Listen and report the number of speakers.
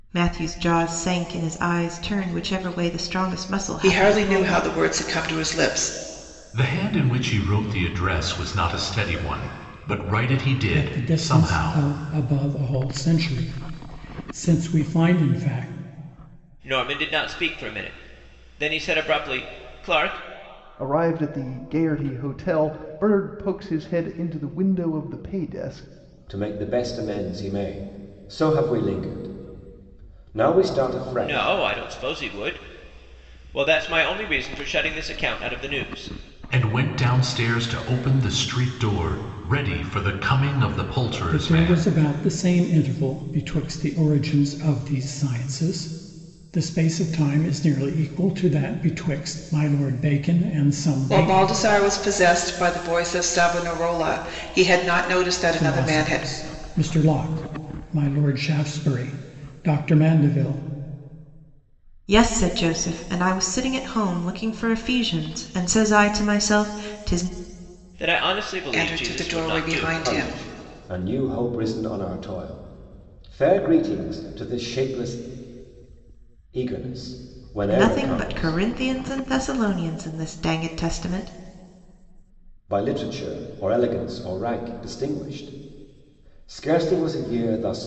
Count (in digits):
7